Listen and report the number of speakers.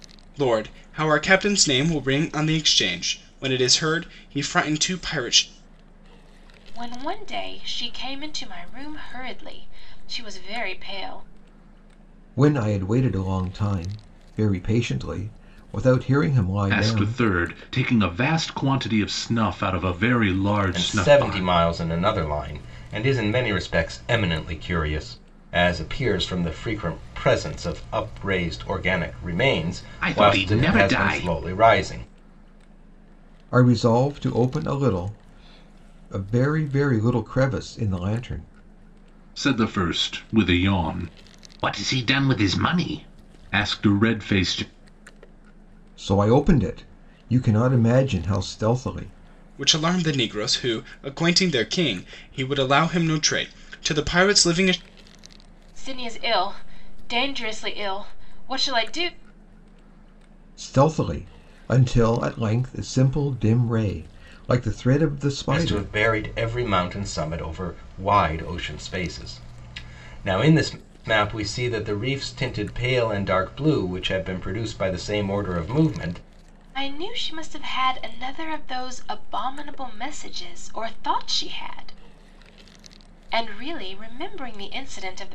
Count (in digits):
5